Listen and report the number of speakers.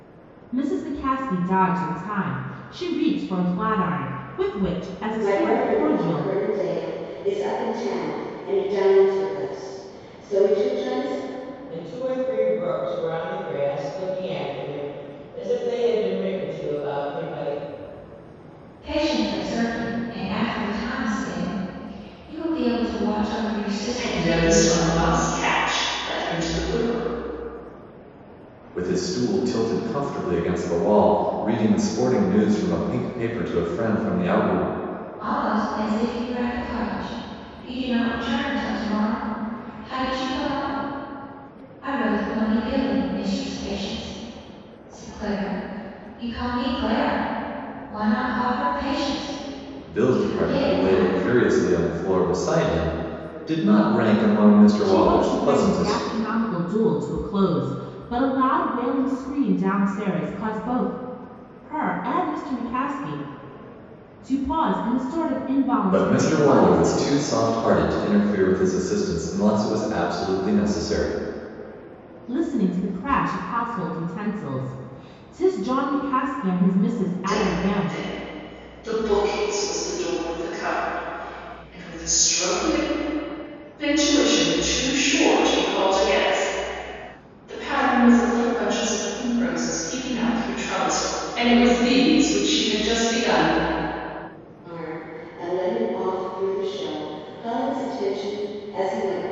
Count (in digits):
6